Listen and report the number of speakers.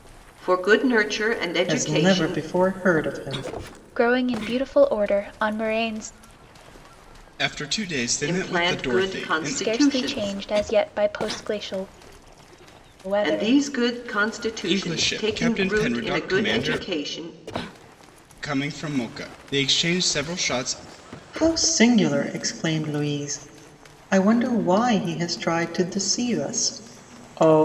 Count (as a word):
four